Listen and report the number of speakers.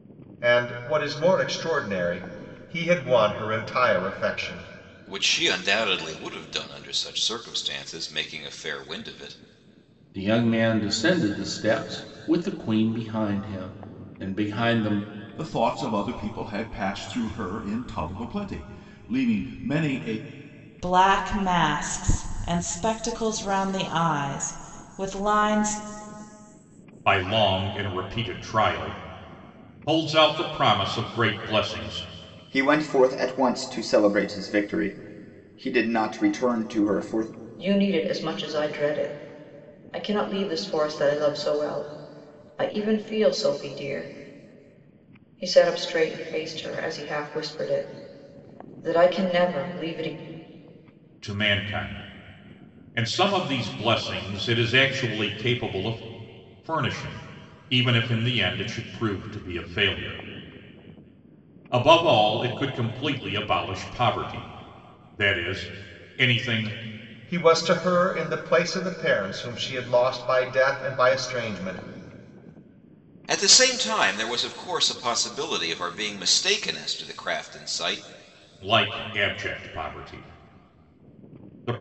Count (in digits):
8